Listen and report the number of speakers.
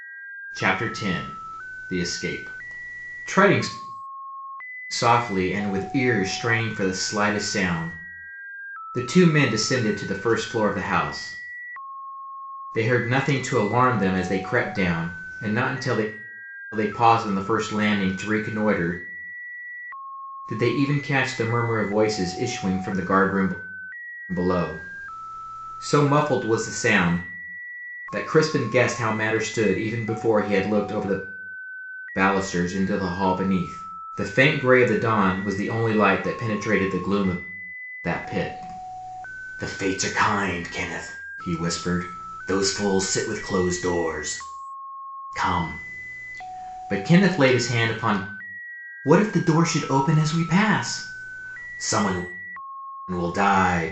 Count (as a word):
one